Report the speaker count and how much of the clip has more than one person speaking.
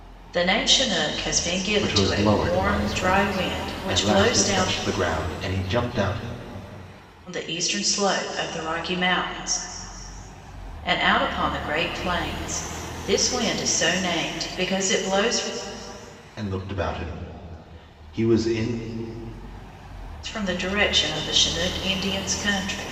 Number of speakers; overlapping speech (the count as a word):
two, about 11%